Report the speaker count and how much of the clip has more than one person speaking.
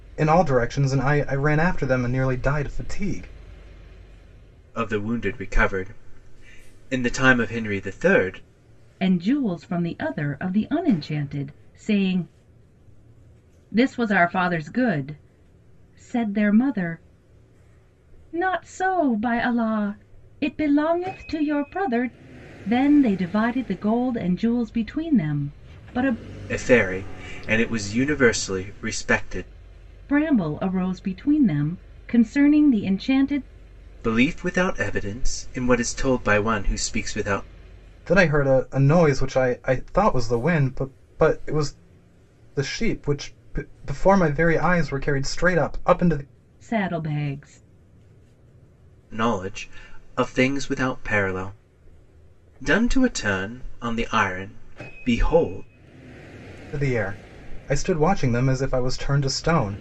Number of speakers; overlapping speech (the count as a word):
three, no overlap